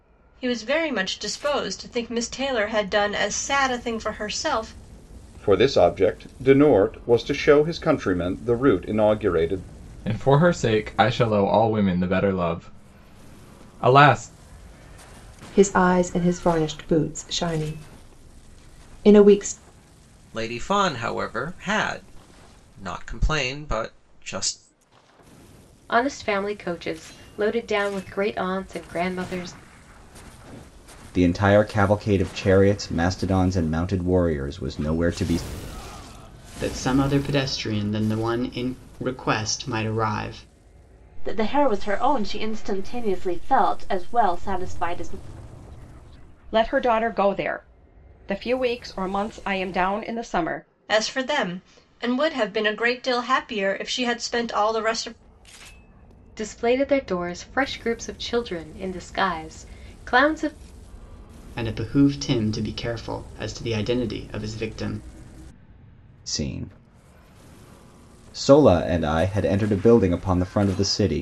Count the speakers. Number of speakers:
10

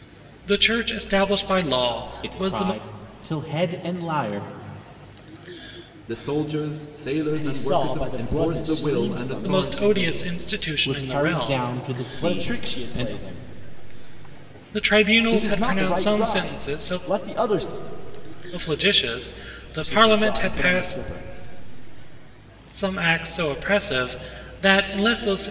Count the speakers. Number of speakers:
4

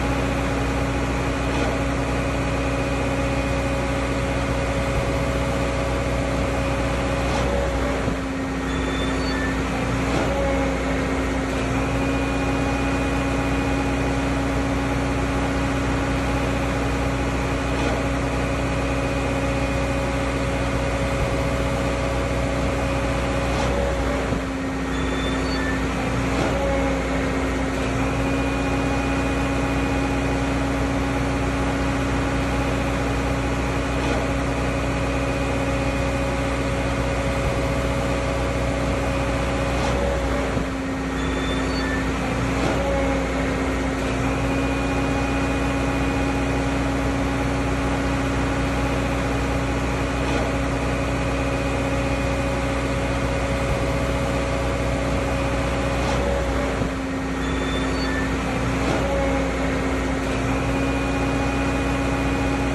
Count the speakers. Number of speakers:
0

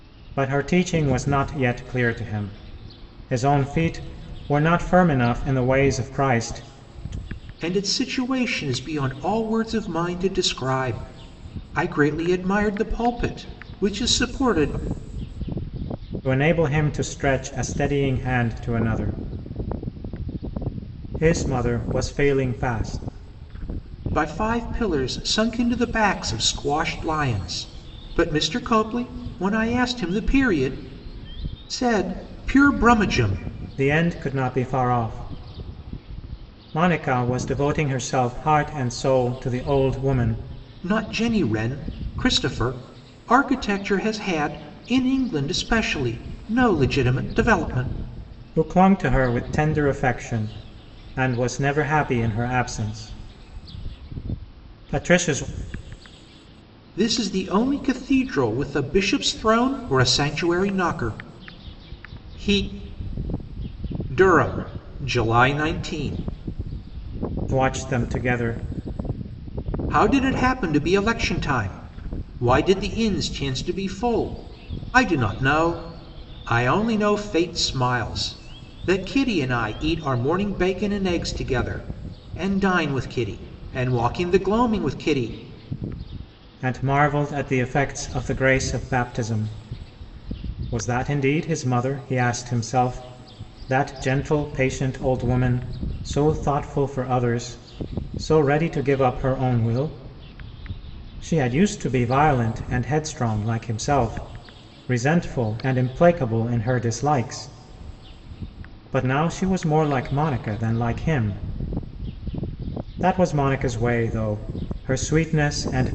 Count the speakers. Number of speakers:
2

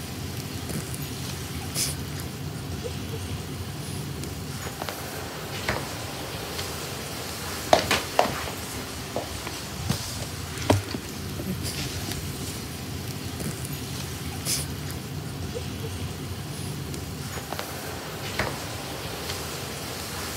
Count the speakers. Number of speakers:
0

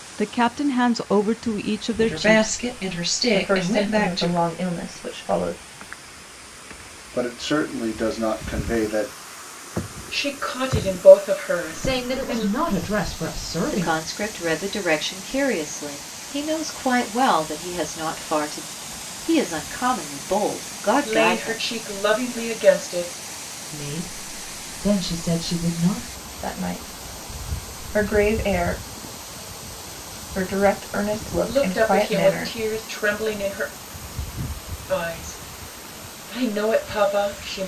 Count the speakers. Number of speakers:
7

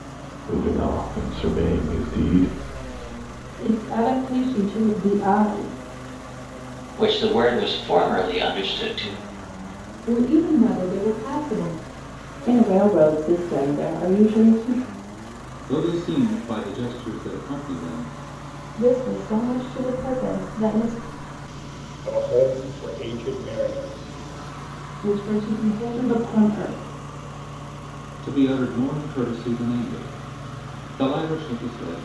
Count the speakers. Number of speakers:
8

